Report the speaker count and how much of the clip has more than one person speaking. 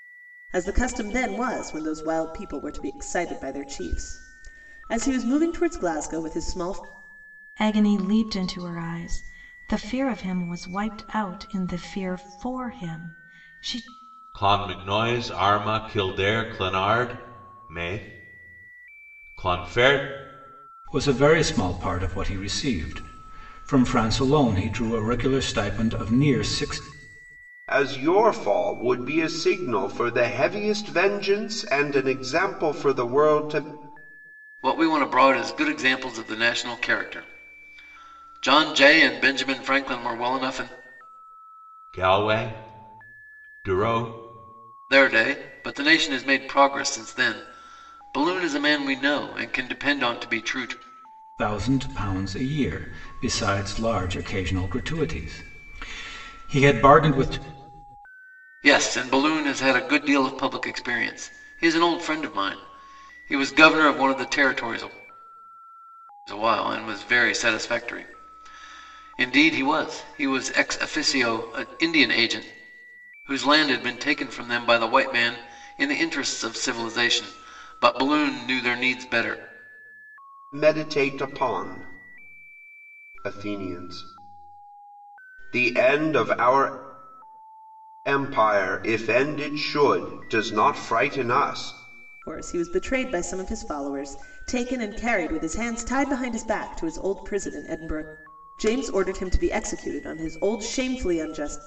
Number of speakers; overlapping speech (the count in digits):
6, no overlap